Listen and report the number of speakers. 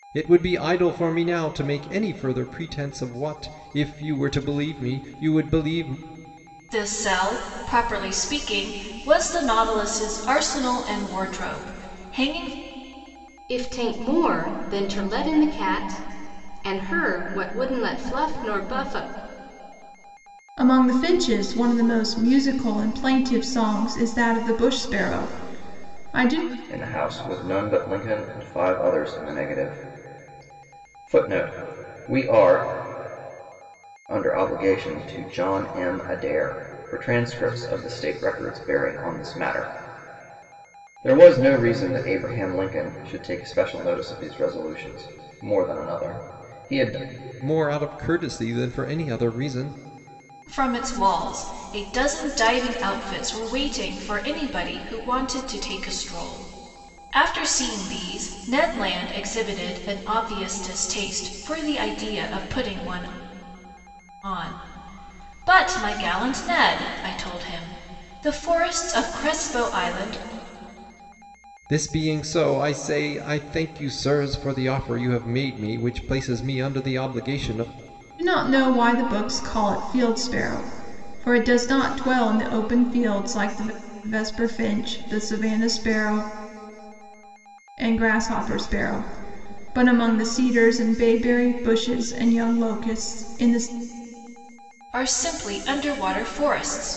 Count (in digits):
5